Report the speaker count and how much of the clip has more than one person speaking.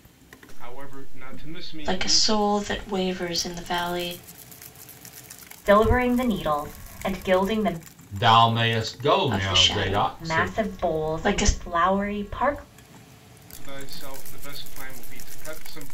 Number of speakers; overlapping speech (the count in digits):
4, about 18%